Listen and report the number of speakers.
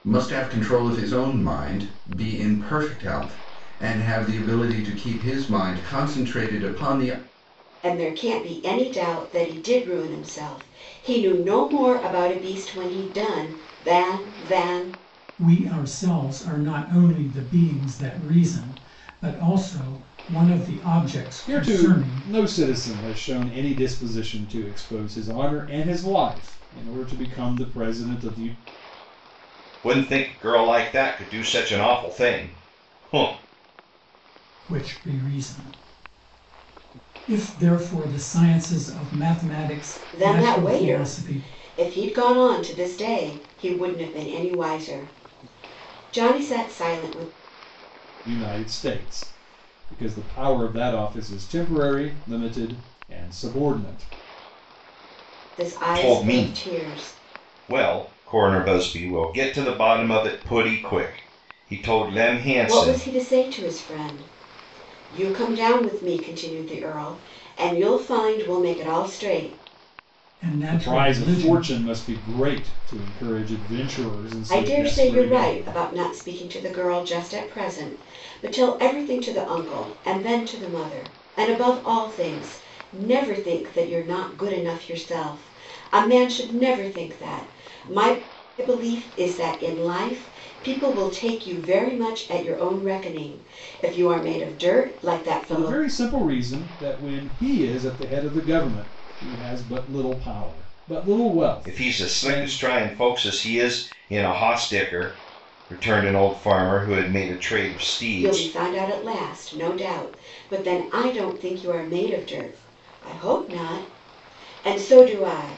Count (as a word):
five